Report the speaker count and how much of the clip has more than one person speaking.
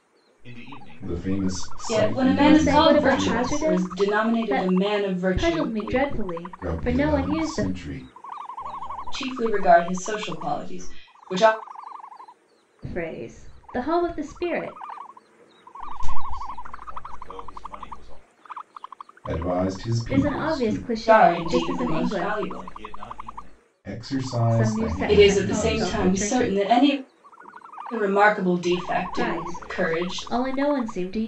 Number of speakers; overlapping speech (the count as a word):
four, about 45%